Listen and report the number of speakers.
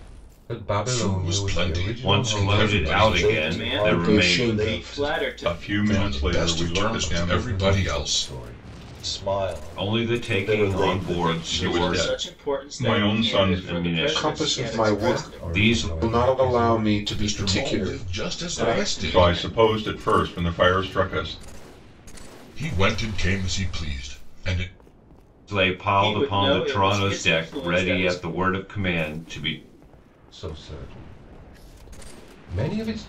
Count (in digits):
7